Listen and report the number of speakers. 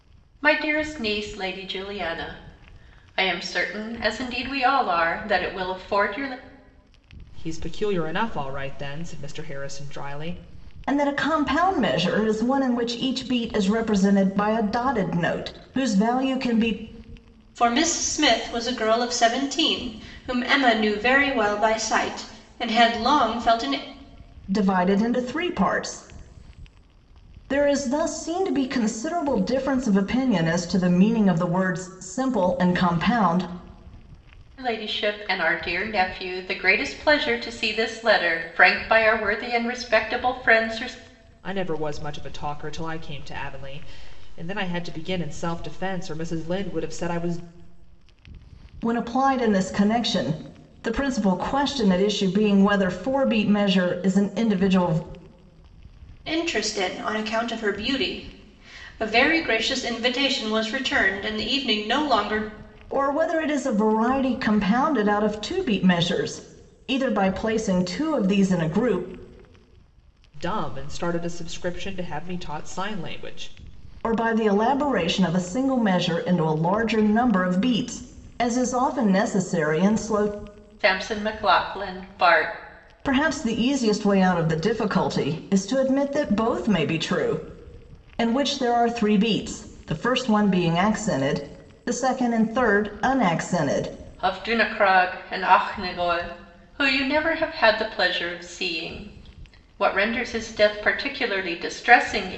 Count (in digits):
4